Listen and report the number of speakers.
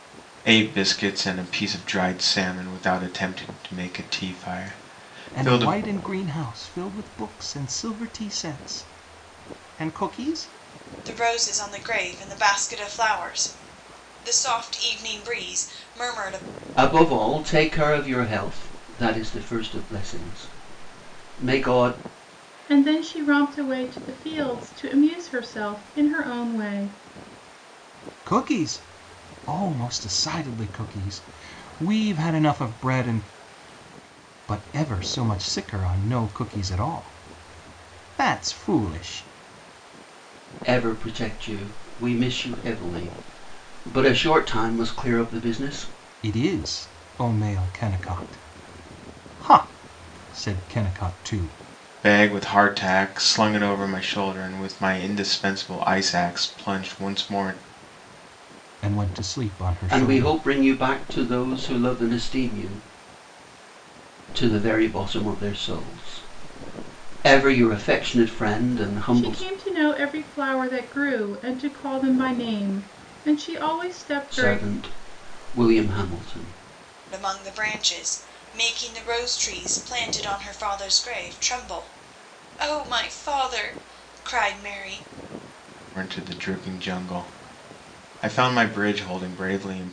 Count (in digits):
5